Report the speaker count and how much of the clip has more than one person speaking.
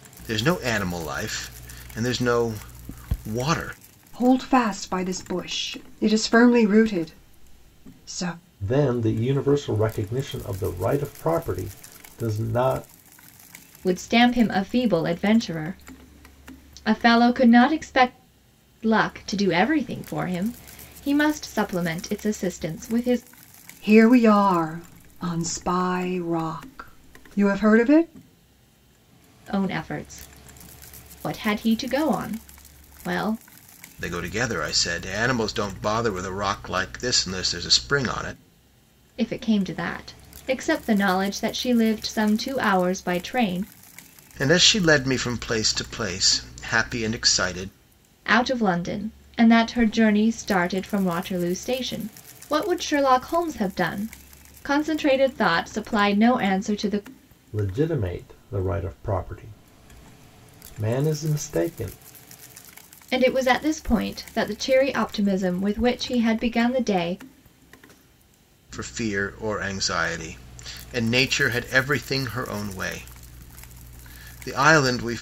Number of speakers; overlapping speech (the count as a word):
four, no overlap